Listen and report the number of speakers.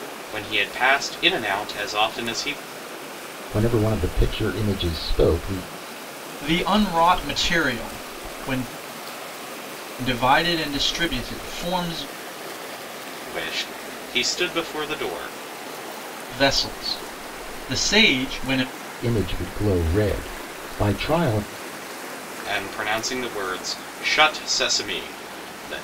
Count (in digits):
3